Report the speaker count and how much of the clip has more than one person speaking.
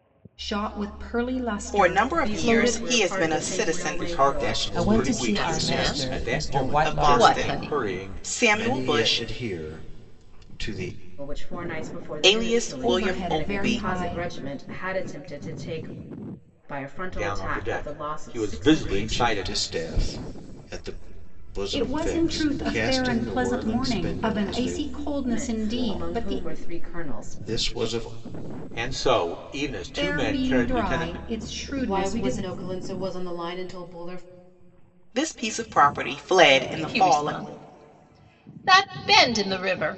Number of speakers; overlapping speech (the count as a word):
seven, about 49%